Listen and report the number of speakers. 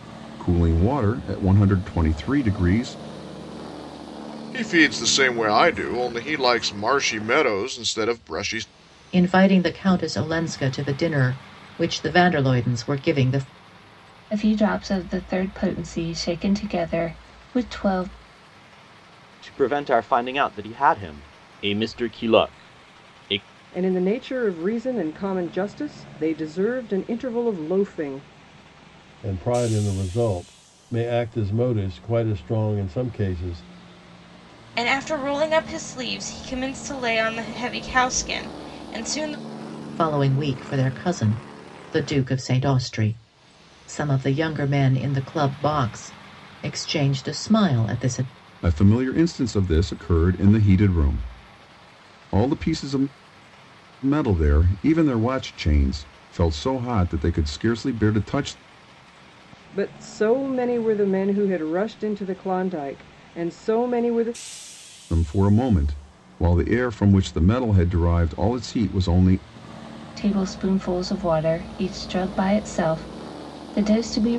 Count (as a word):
eight